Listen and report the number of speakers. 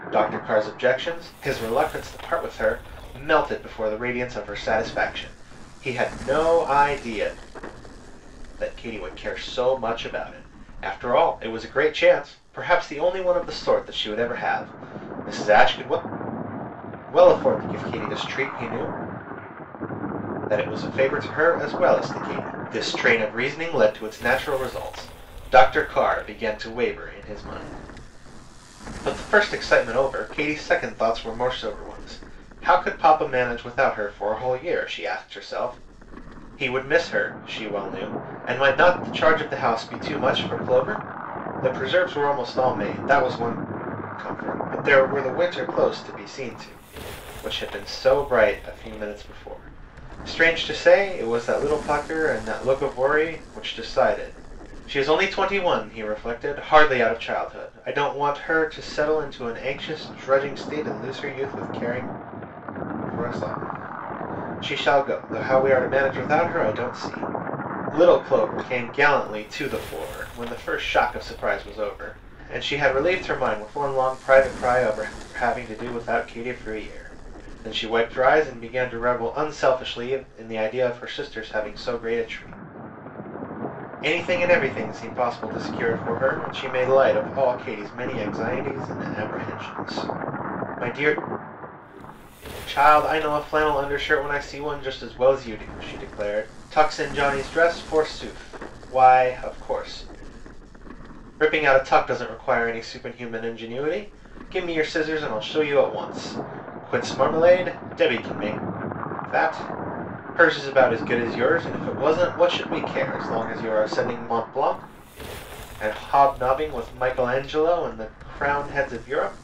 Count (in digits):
1